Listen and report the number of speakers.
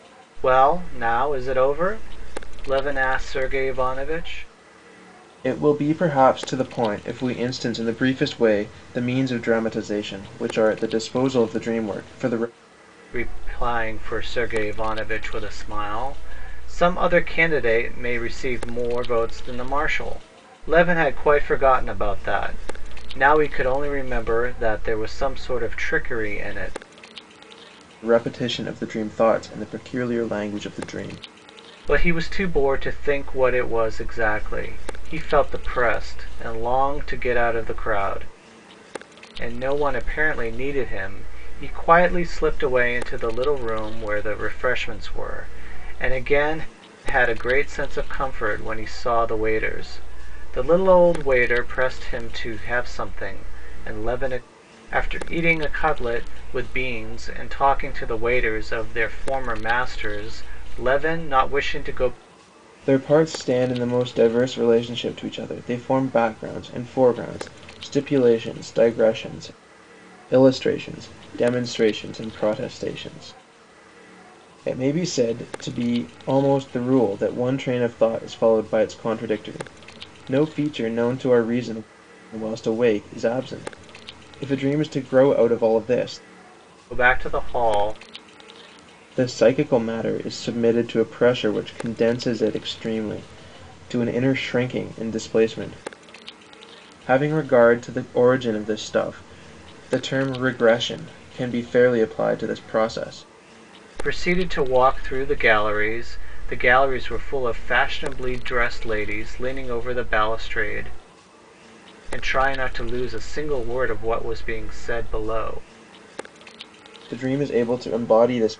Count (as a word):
two